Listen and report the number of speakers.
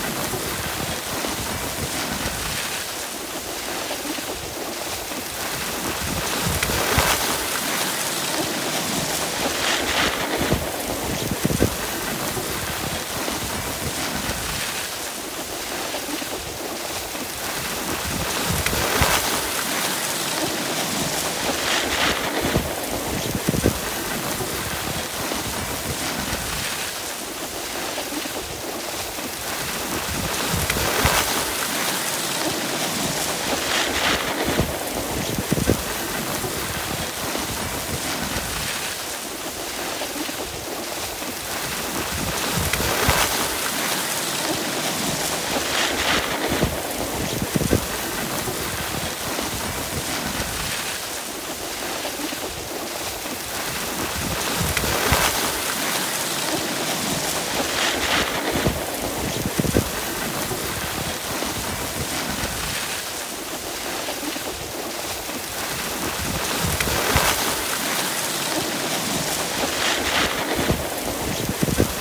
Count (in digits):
0